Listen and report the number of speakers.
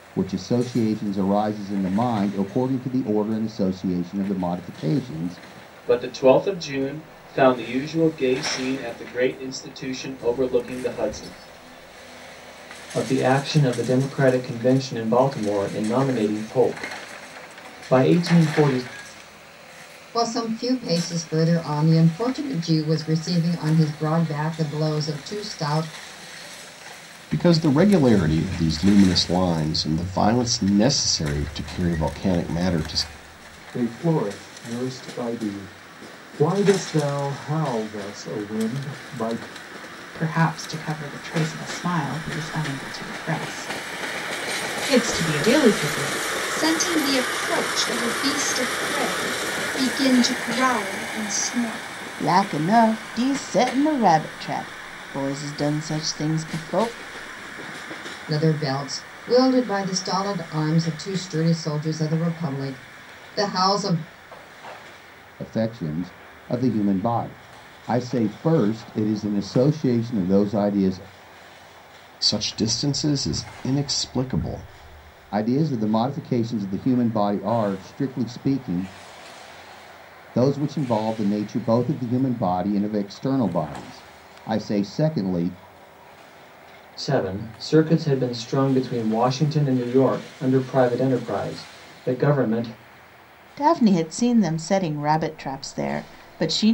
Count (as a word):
nine